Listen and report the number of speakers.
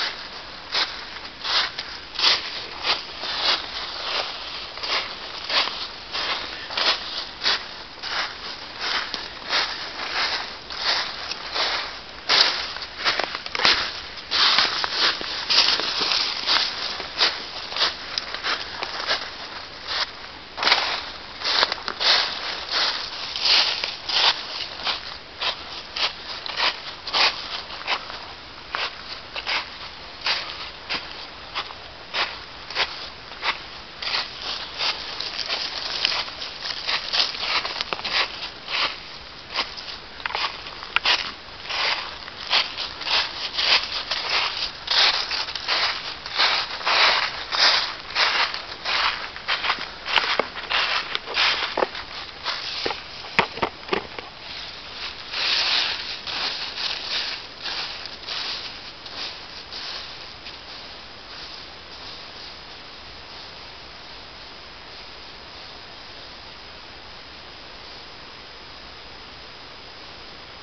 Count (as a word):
zero